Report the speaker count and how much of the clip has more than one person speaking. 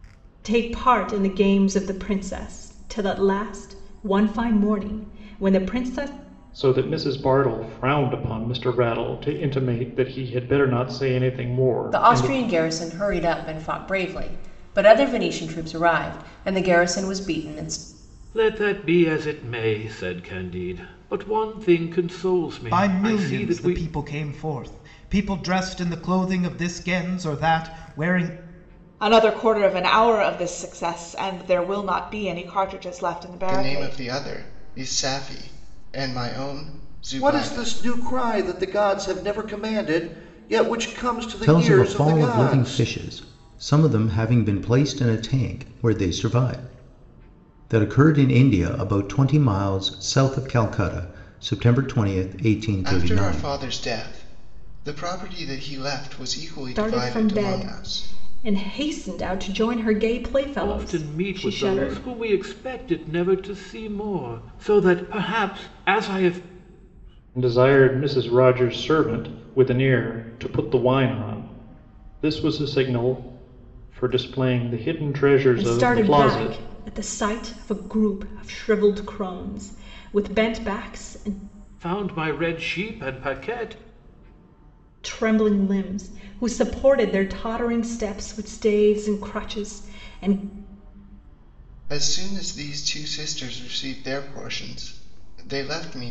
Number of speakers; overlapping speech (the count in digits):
9, about 10%